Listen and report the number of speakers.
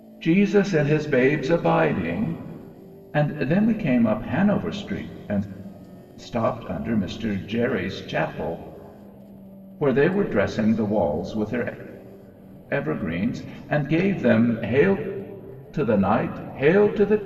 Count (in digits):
1